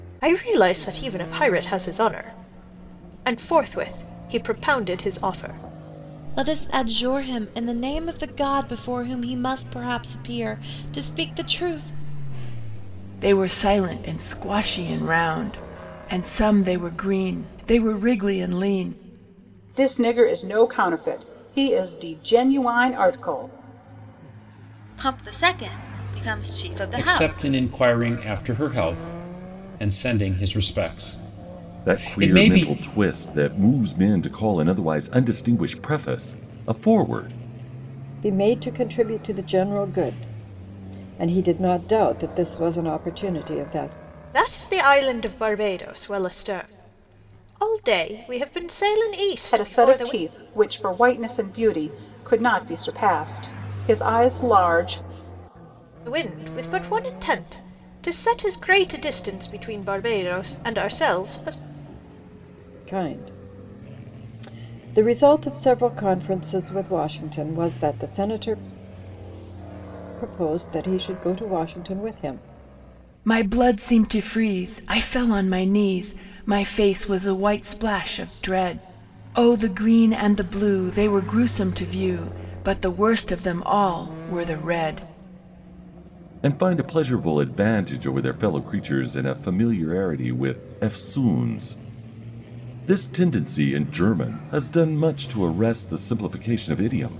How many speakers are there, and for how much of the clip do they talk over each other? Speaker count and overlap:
8, about 2%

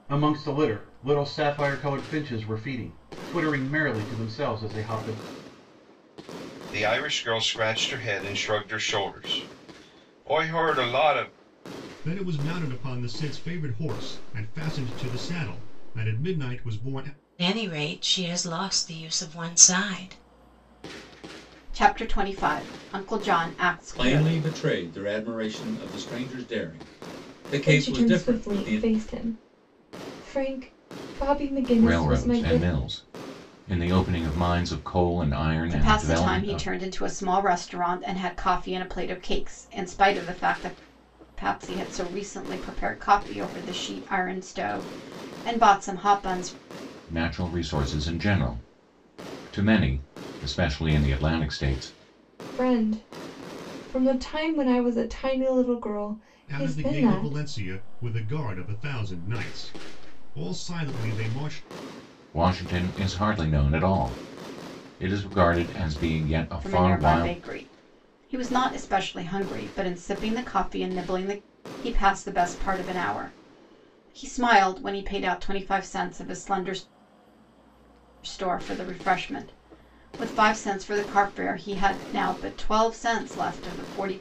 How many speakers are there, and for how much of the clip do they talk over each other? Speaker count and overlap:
8, about 7%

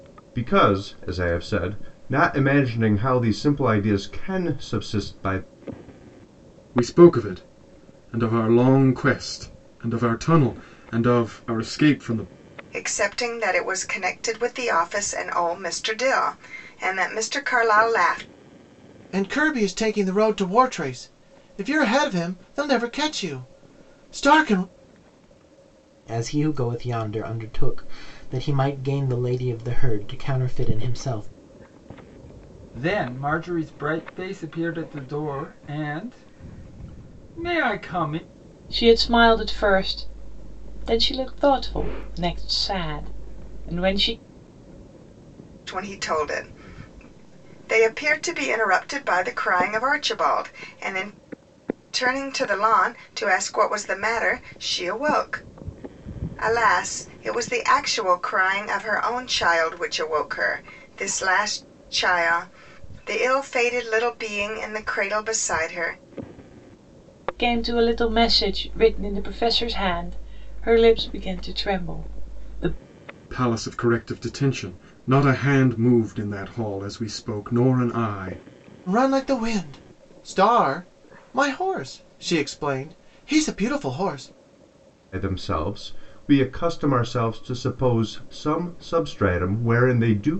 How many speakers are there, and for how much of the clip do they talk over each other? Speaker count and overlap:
7, no overlap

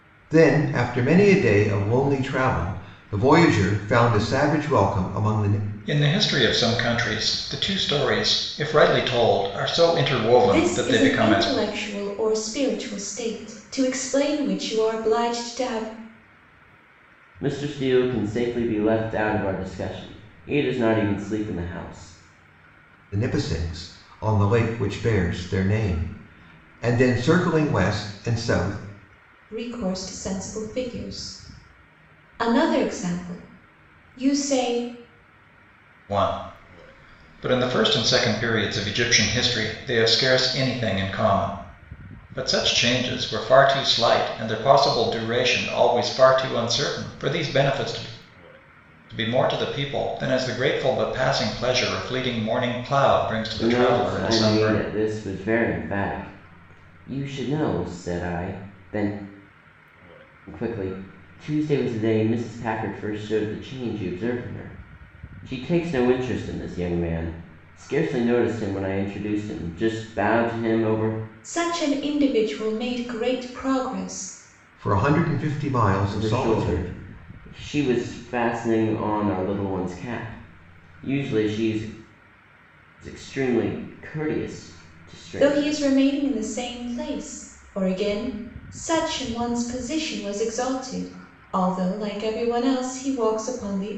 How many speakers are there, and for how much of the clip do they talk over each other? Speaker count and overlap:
4, about 4%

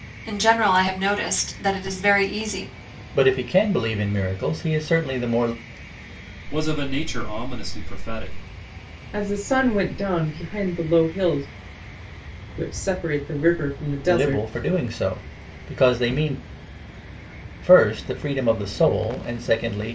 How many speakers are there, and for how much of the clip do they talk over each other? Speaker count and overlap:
4, about 2%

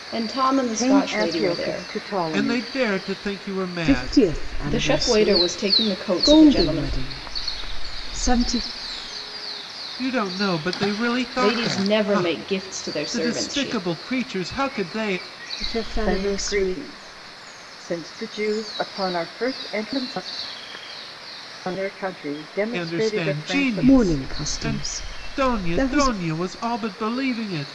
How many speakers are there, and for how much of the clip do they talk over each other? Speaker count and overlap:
4, about 33%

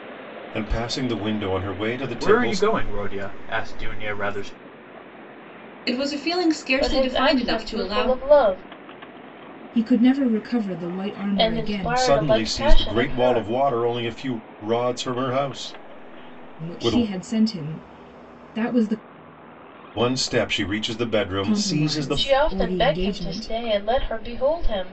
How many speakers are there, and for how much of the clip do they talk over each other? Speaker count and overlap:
5, about 27%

